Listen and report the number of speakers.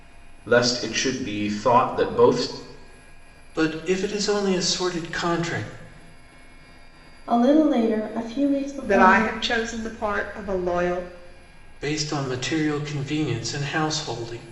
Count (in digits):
4